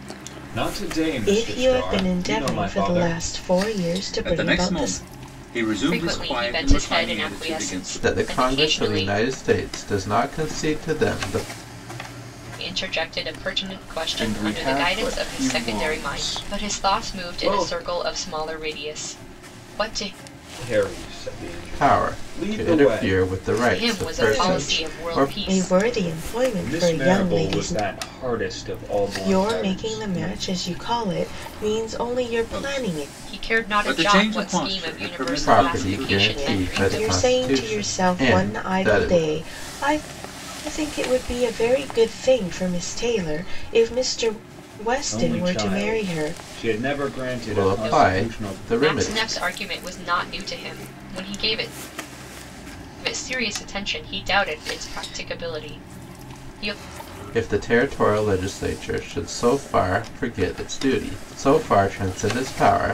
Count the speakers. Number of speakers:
5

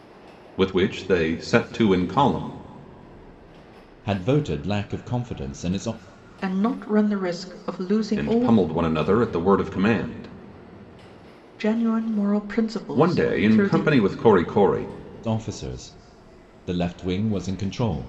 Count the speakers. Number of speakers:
3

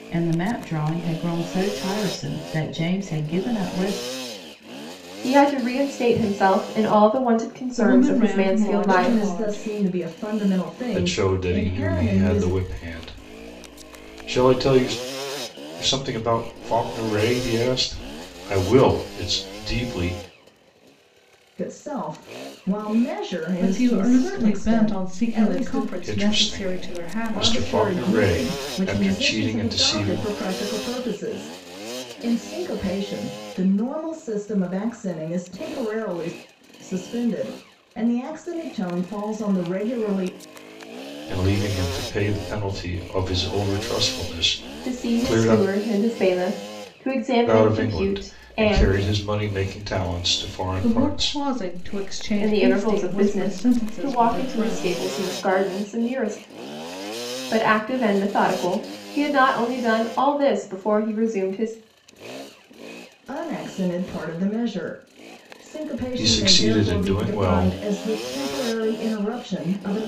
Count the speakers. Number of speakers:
5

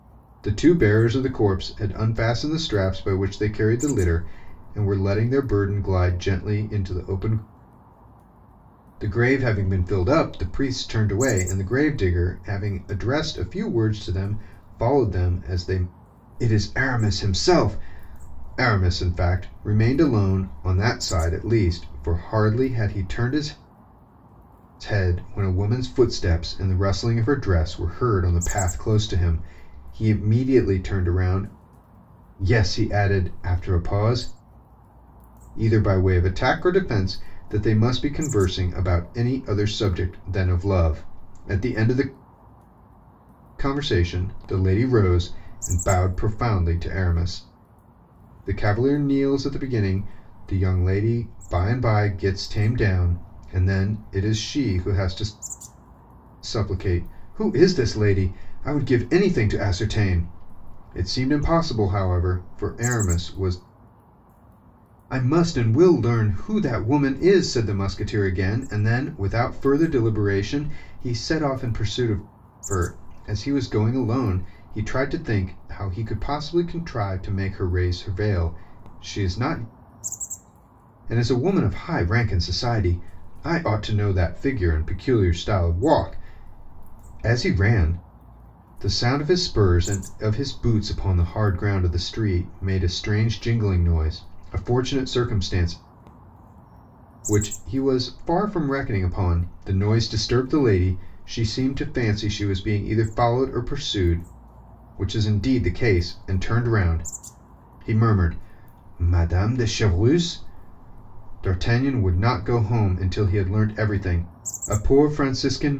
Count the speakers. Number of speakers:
1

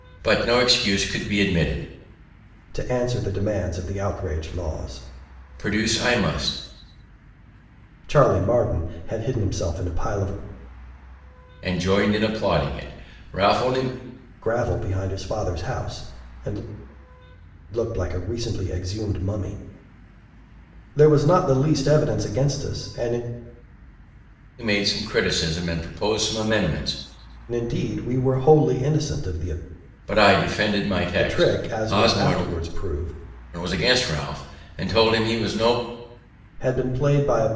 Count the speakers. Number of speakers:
2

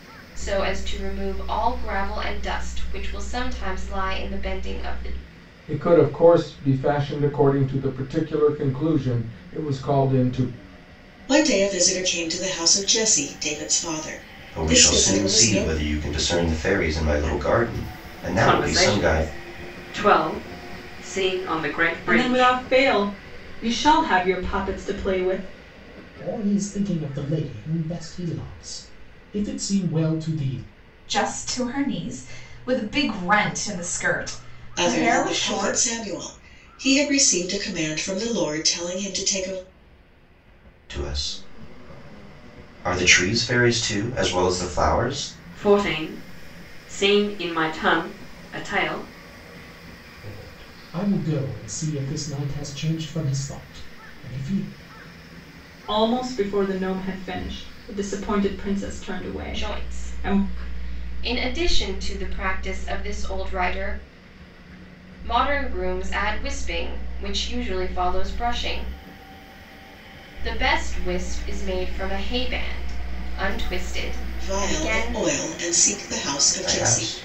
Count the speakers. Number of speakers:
8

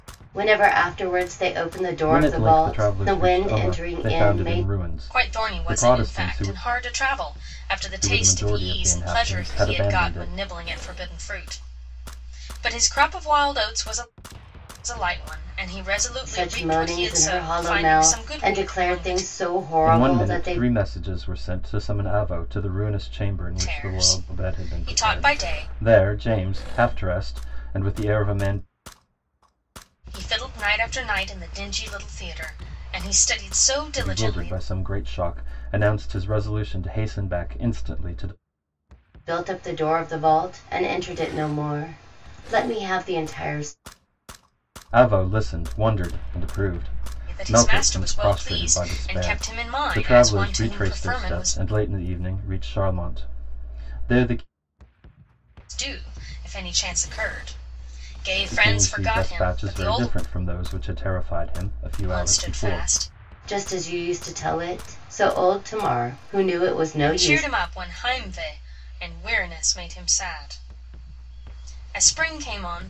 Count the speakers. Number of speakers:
3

